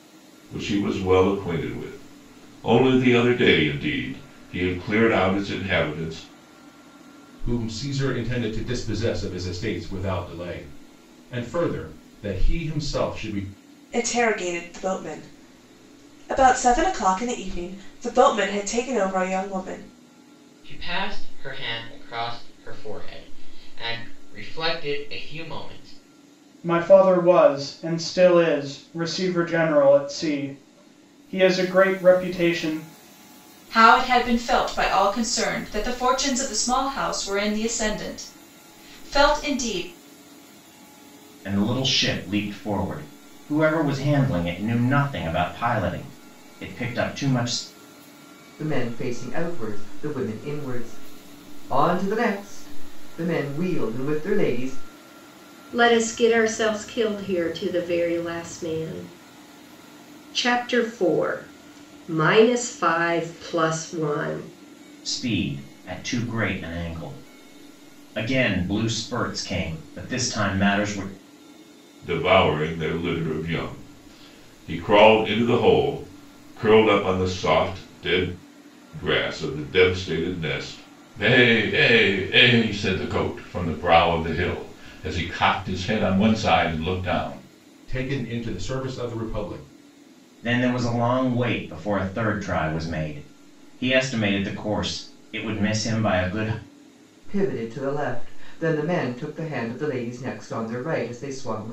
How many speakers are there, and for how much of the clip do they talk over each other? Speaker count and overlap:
nine, no overlap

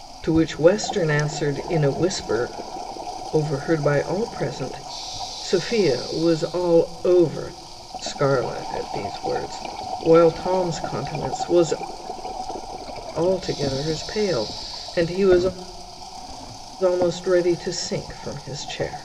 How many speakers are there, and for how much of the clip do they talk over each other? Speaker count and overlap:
one, no overlap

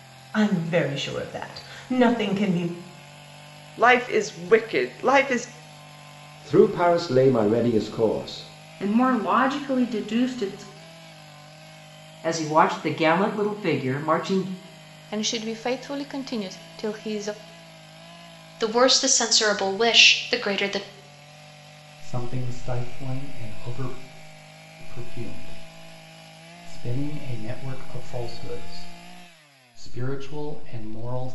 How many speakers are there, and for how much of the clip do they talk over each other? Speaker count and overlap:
eight, no overlap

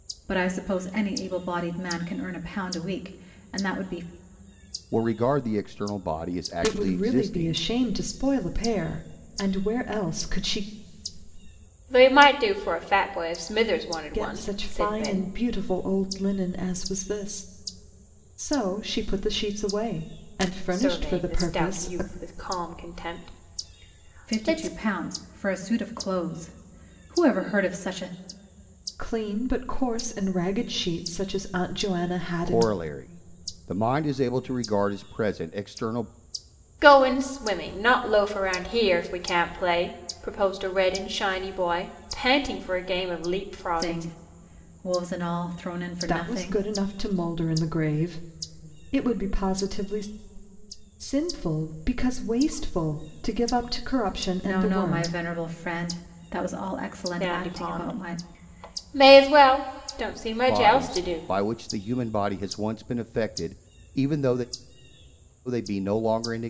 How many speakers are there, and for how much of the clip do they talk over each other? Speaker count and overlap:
four, about 12%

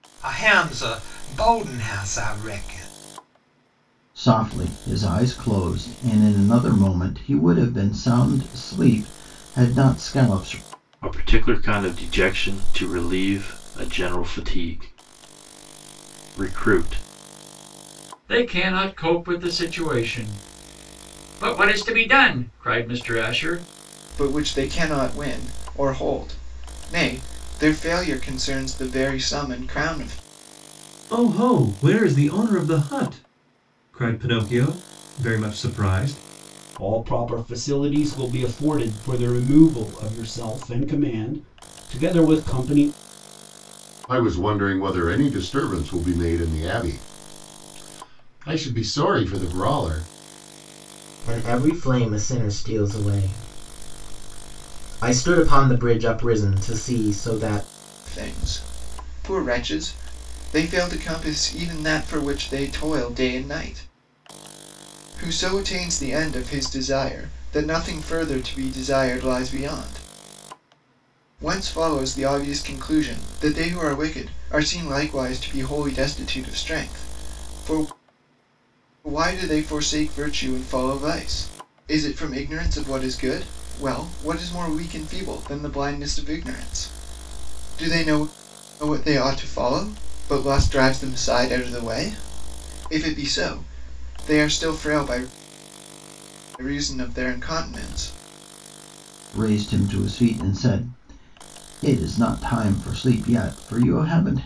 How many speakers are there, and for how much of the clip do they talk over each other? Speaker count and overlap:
nine, no overlap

